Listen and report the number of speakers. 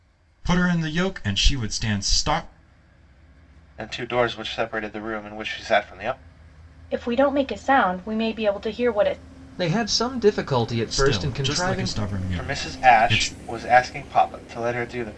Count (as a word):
four